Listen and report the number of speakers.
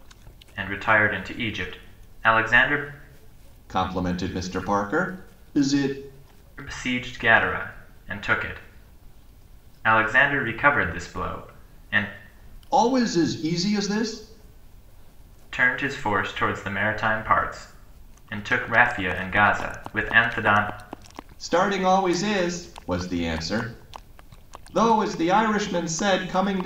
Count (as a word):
two